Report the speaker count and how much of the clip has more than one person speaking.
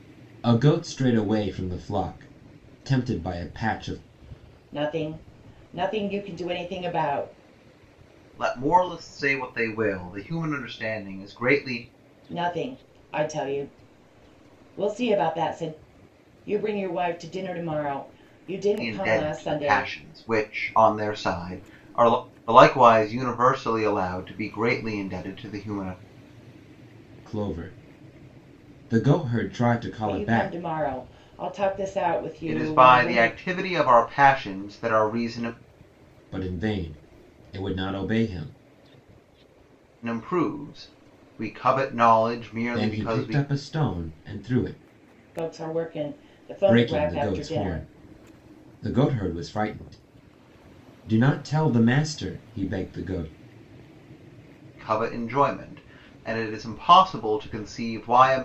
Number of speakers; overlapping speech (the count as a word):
three, about 8%